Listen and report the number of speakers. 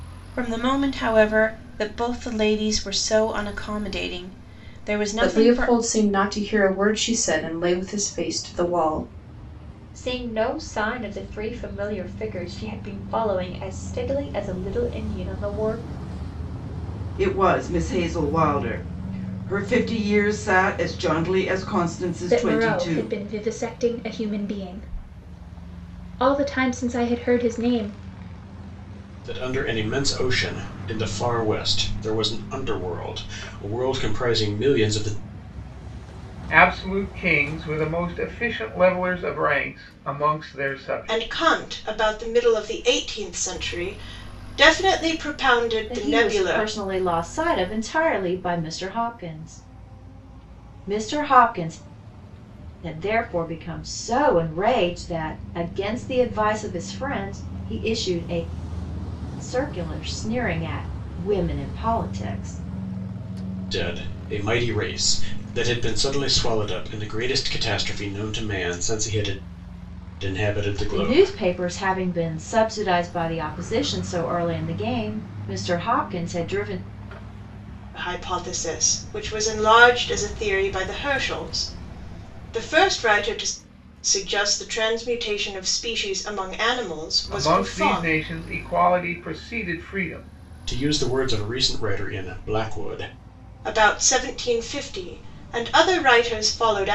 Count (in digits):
9